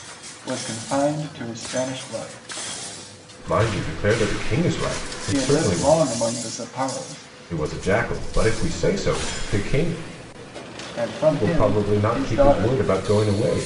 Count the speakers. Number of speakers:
2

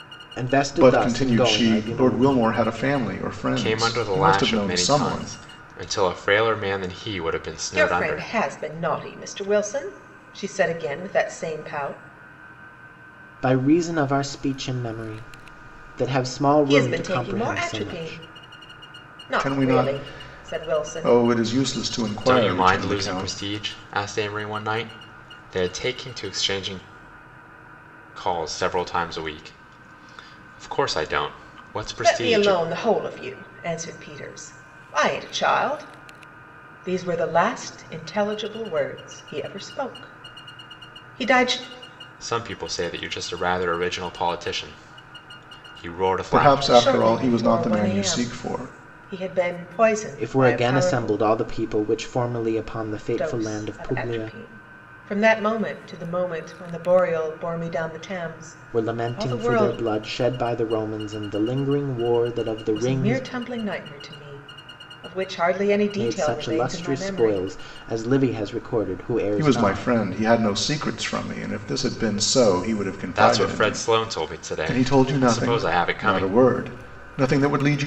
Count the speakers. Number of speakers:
4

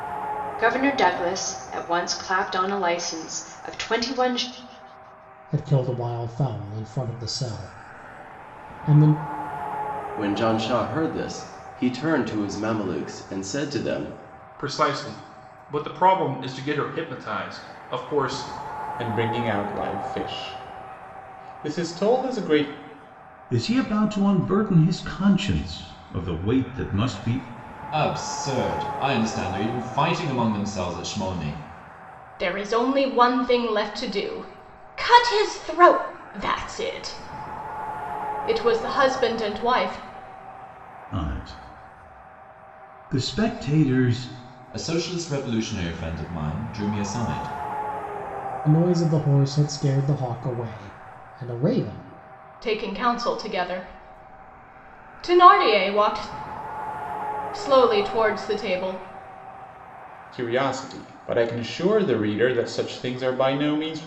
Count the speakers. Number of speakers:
8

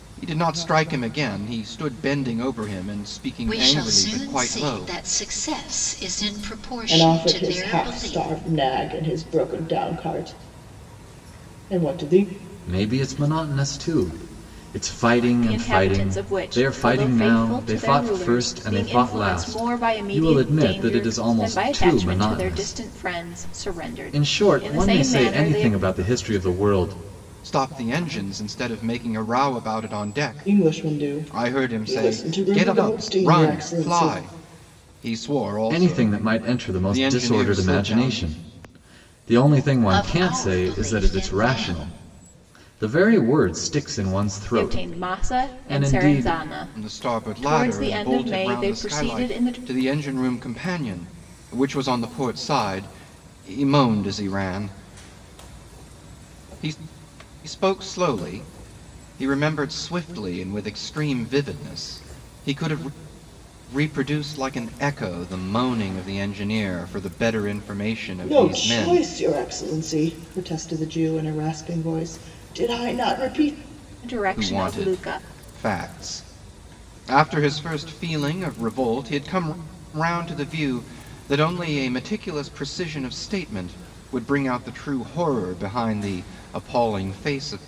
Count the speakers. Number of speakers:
5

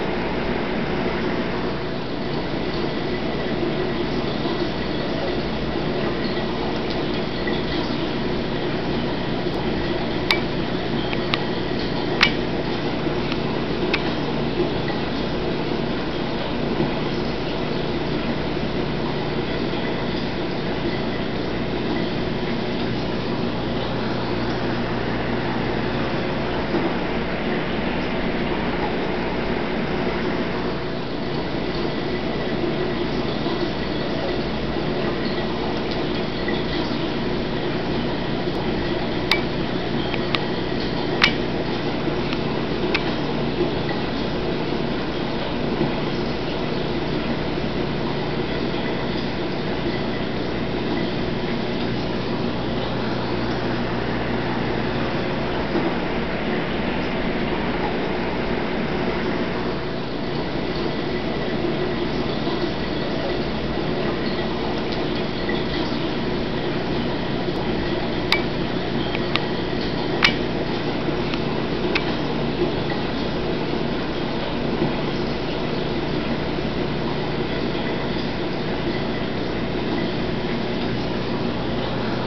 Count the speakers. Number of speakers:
0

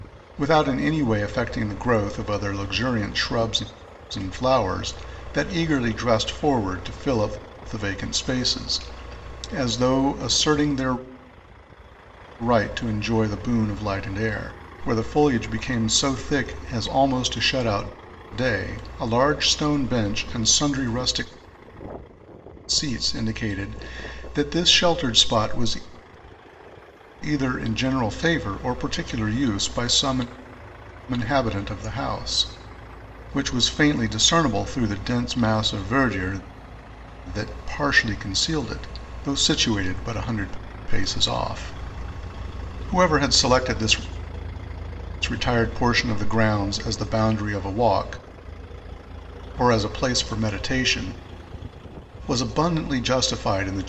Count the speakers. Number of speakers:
1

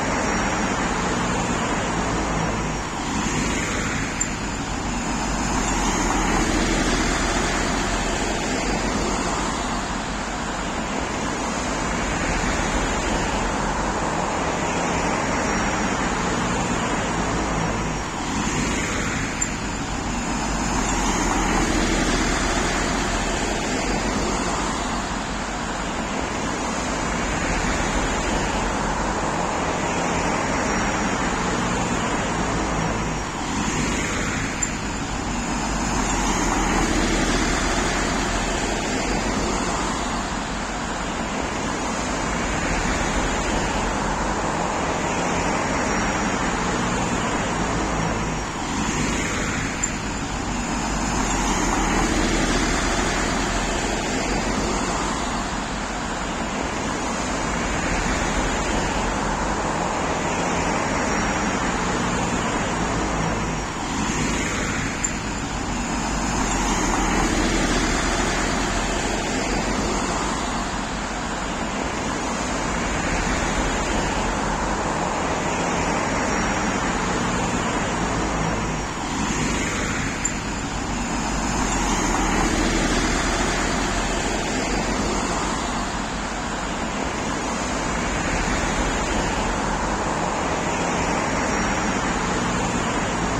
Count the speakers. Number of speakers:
0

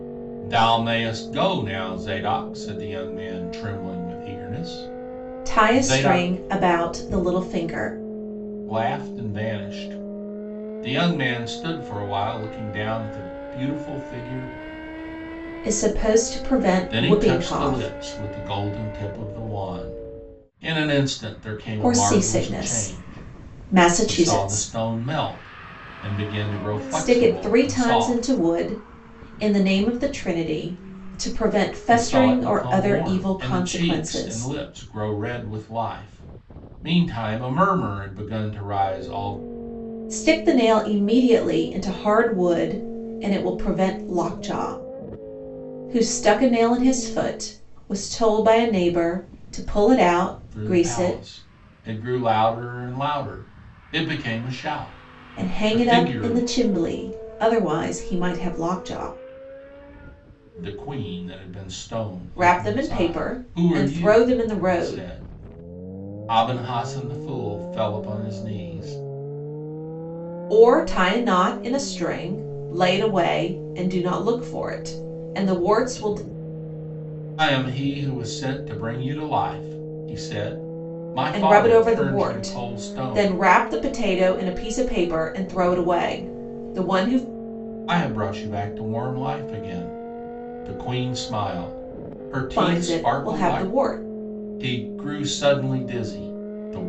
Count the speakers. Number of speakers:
2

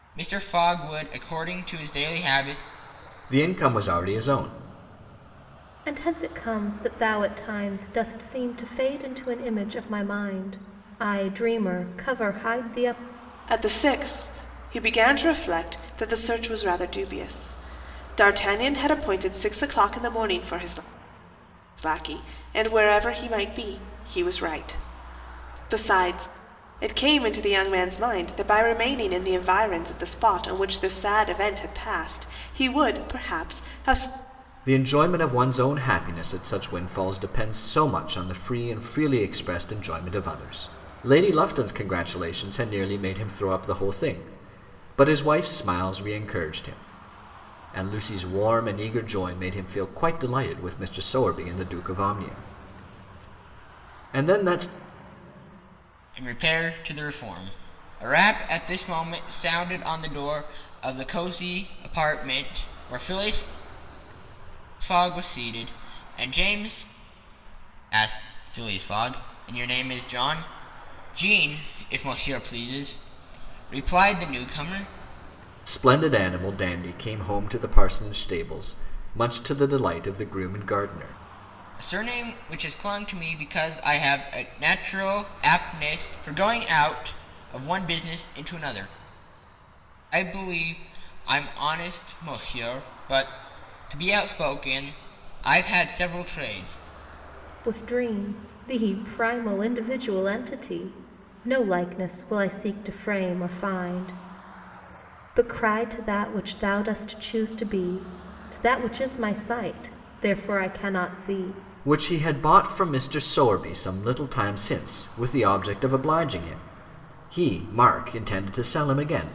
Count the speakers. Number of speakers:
4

